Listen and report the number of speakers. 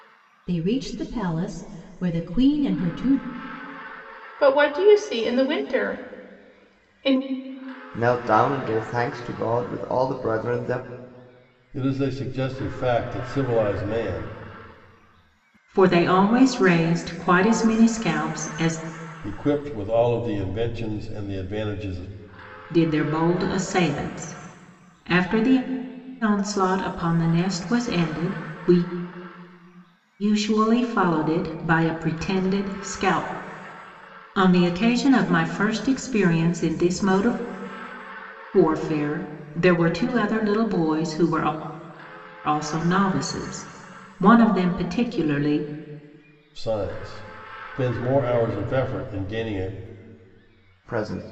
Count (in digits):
5